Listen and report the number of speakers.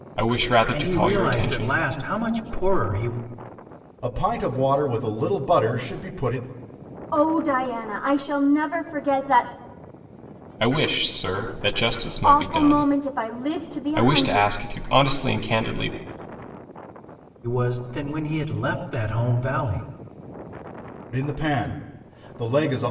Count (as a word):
four